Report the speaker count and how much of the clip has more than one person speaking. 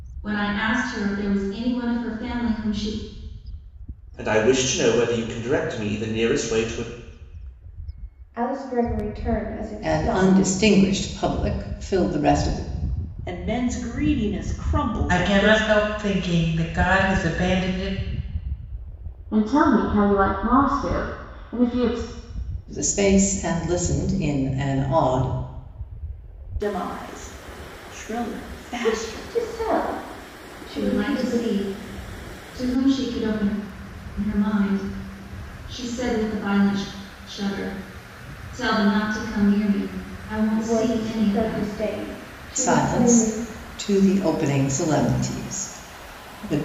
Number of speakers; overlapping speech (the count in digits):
7, about 9%